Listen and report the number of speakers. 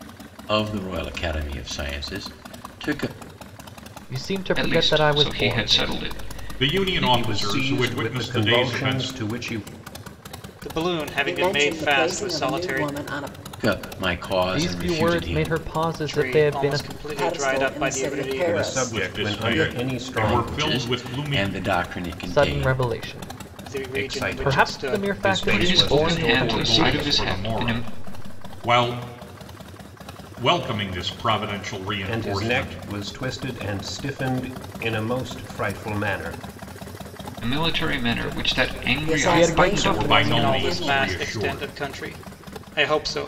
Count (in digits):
7